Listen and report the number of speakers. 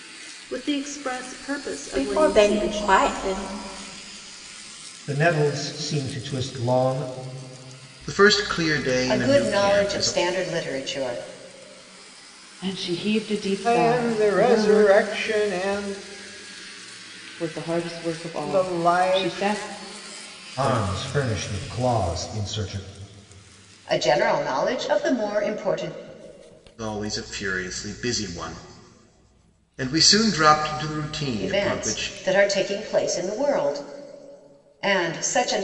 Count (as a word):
seven